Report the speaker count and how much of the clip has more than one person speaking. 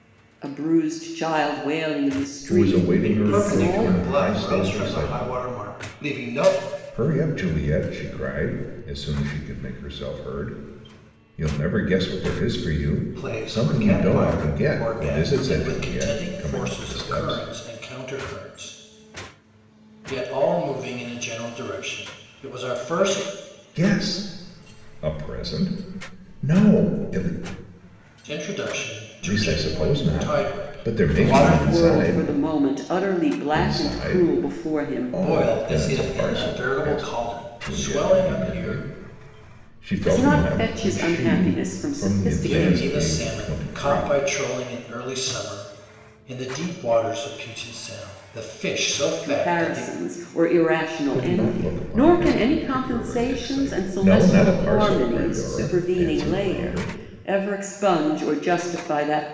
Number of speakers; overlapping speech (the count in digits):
3, about 44%